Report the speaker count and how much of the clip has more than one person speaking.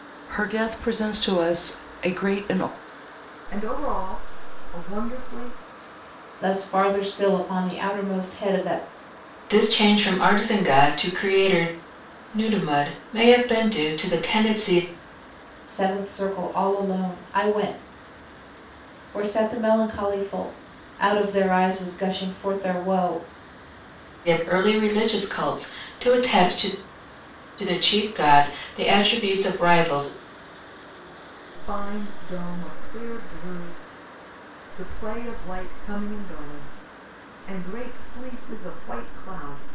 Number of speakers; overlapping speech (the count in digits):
4, no overlap